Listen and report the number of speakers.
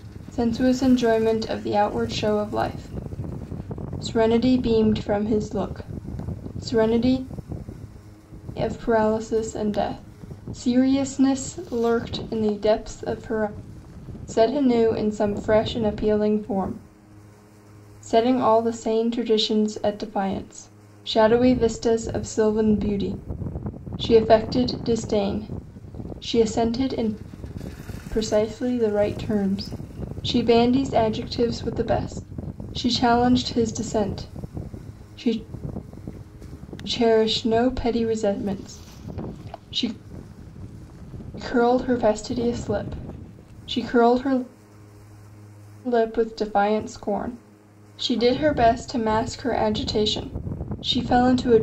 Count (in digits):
1